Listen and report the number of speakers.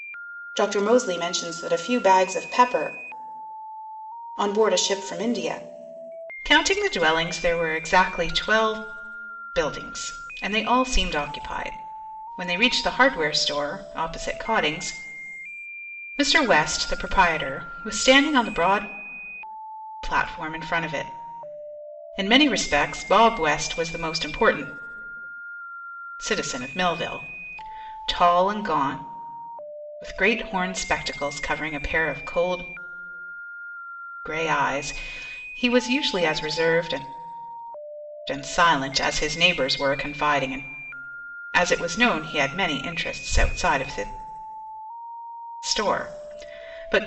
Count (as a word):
one